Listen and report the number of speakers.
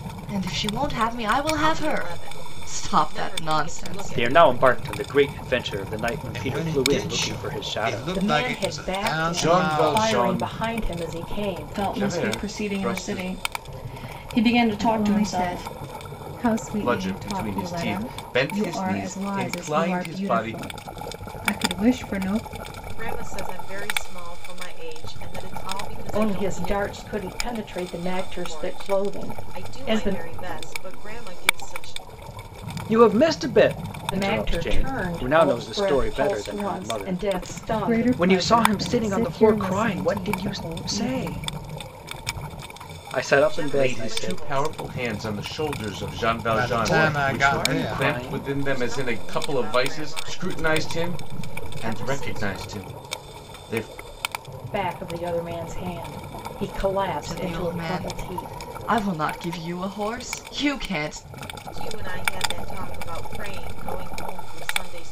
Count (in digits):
8